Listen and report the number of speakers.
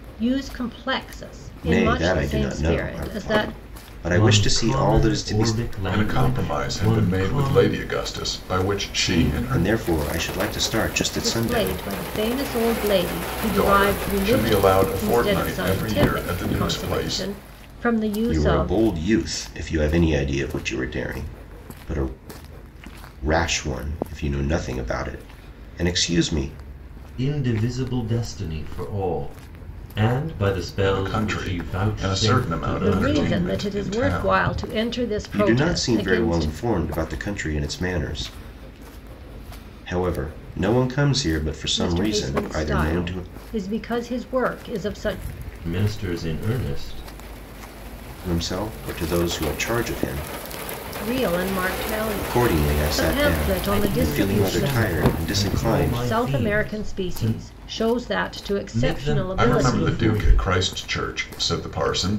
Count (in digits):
4